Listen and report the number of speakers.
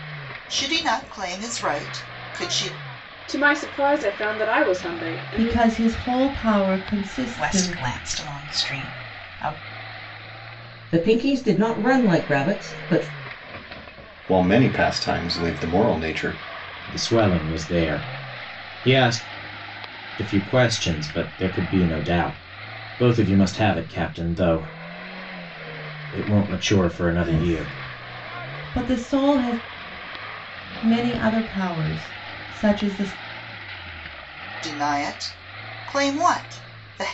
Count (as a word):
seven